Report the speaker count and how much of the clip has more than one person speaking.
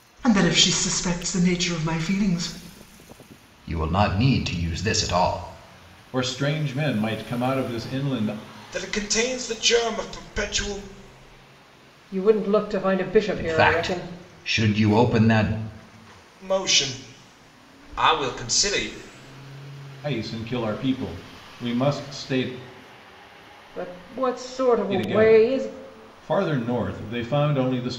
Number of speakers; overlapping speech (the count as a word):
five, about 6%